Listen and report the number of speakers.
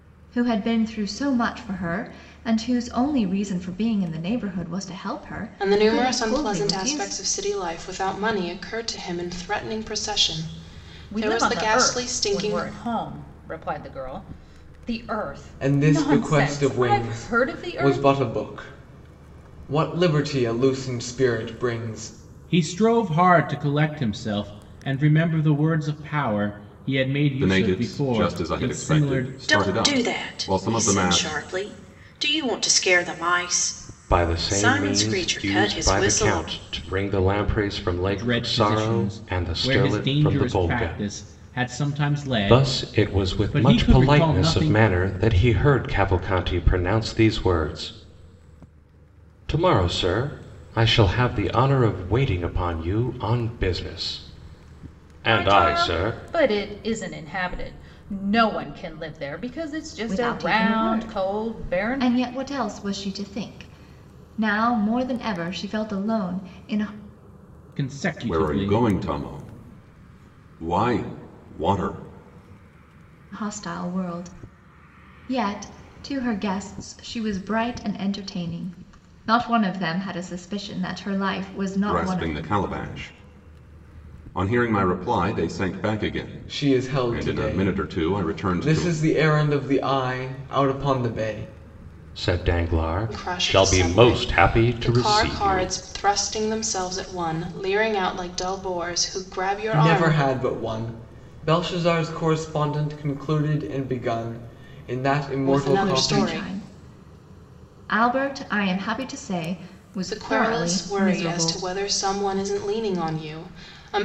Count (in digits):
8